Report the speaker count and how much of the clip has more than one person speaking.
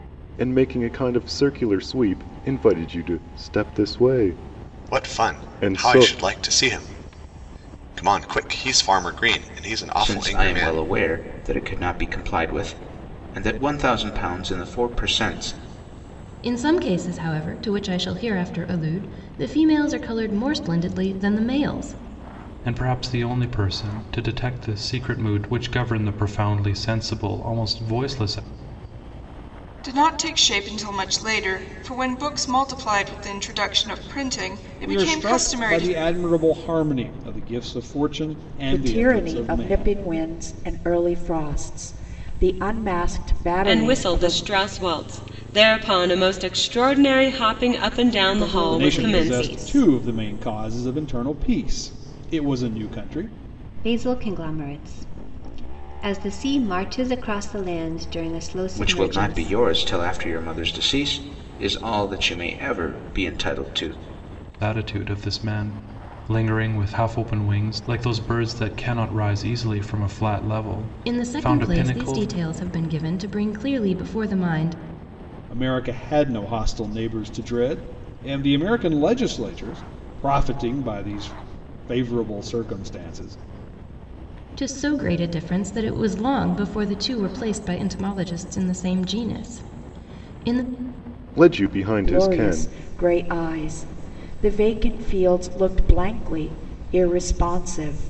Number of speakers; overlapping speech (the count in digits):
10, about 10%